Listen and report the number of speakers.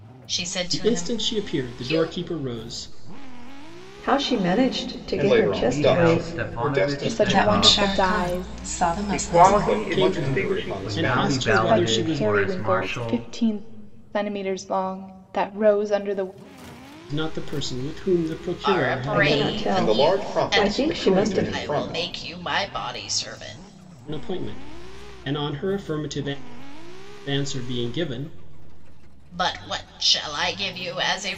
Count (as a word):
eight